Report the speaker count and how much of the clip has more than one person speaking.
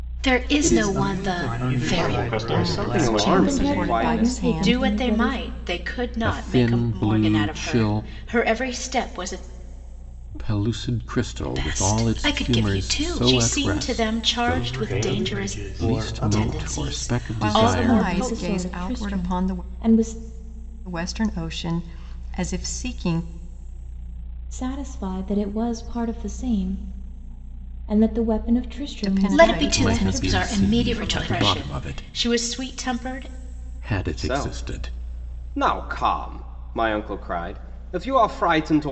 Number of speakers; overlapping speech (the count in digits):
9, about 48%